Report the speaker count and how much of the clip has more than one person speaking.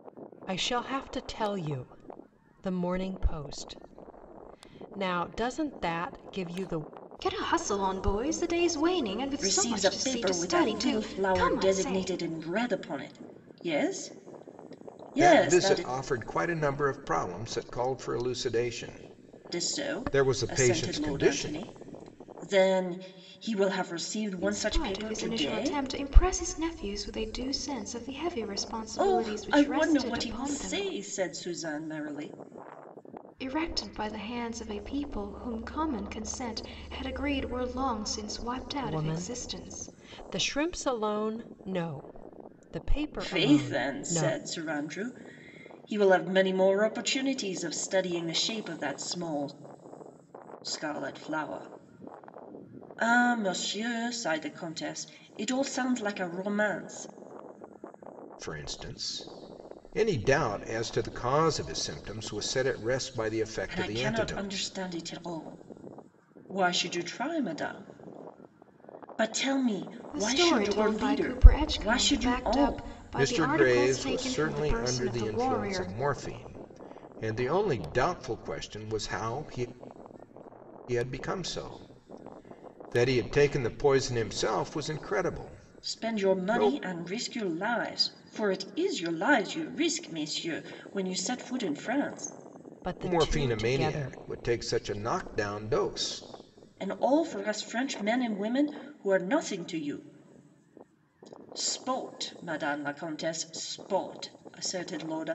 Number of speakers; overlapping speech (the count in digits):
4, about 19%